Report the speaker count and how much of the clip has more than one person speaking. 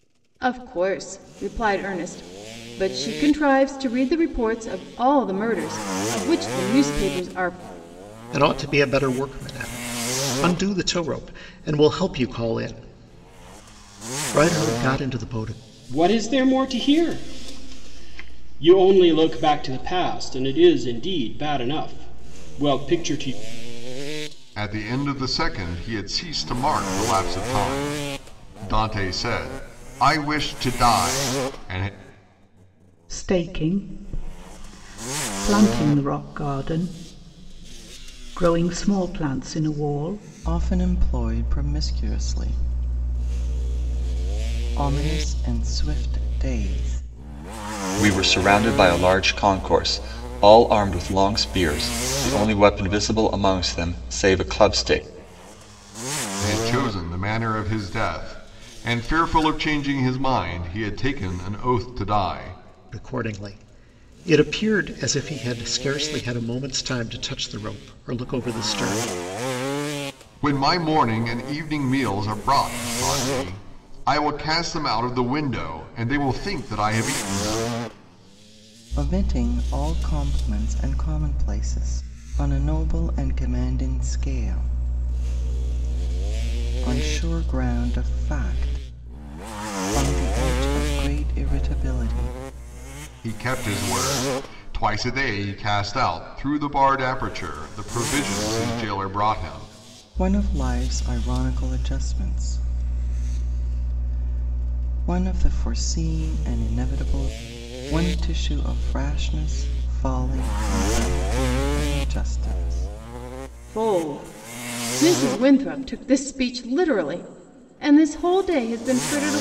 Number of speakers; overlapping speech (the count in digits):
7, no overlap